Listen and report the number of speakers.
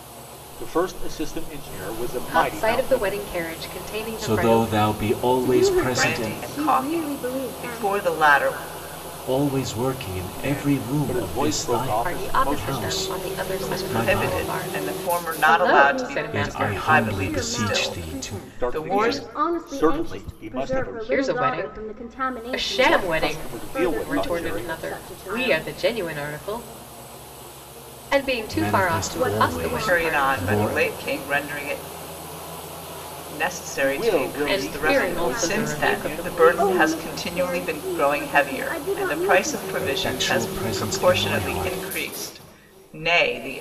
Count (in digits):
5